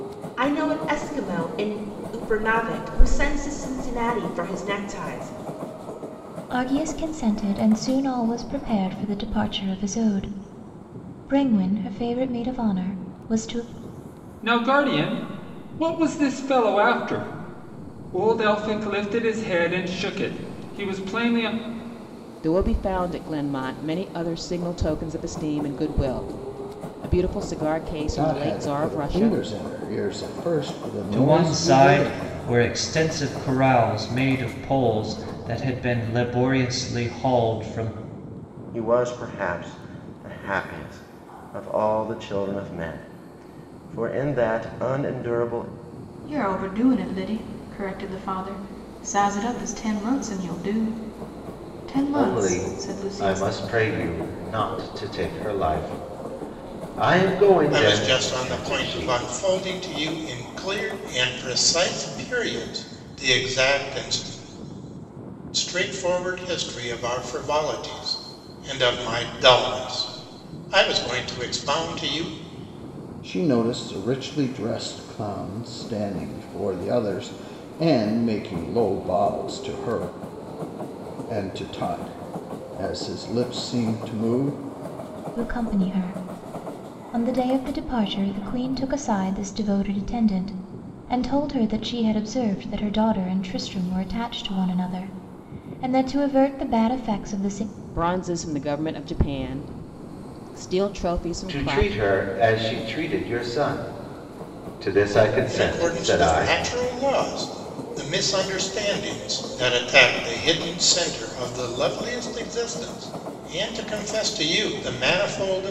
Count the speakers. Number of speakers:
10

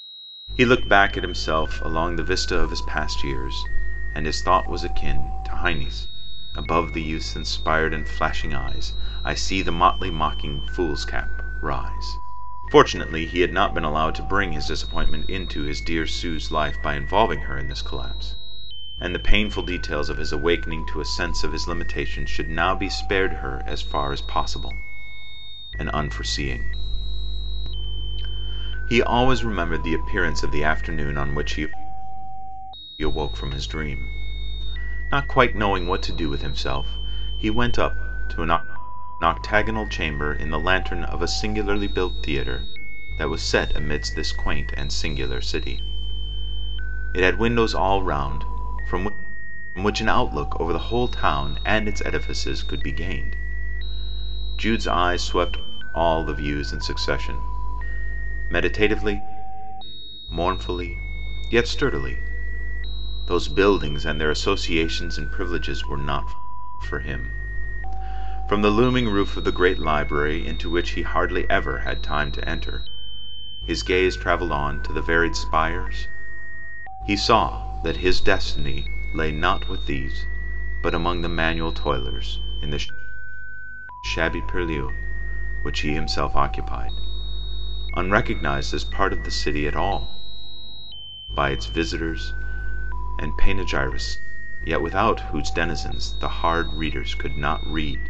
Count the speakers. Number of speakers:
1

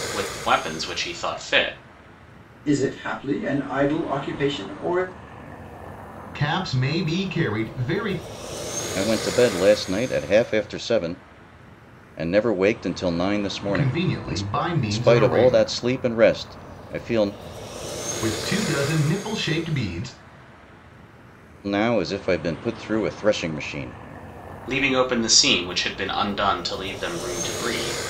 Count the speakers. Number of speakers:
4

